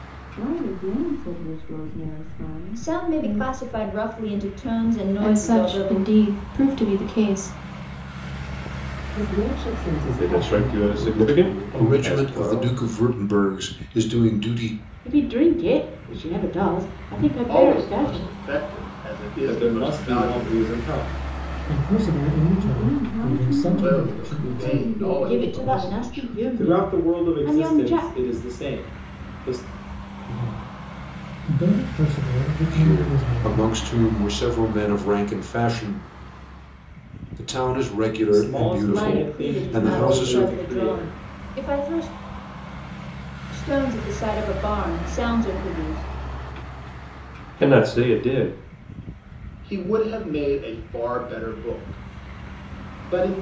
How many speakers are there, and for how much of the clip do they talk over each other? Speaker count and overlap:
10, about 30%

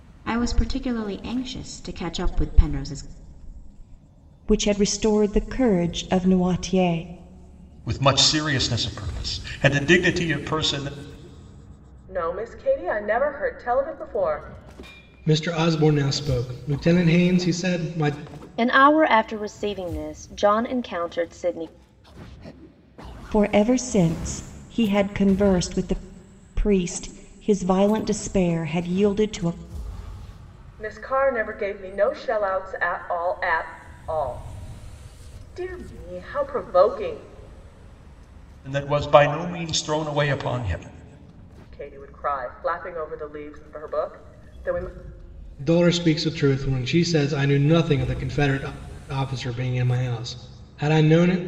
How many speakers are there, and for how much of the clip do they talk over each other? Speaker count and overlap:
6, no overlap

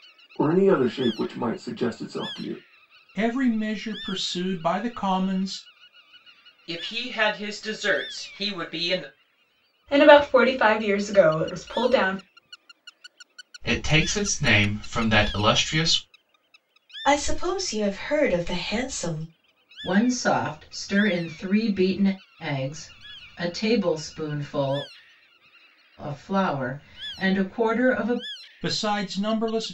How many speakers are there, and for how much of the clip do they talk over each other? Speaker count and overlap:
7, no overlap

